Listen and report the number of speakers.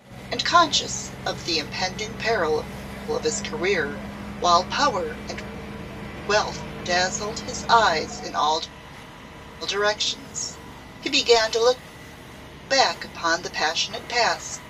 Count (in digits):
1